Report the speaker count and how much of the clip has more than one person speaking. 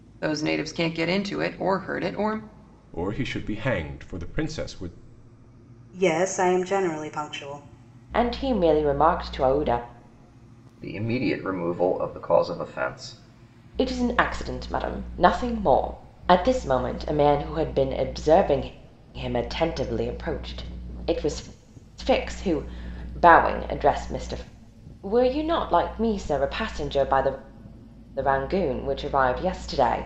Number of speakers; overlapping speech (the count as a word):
five, no overlap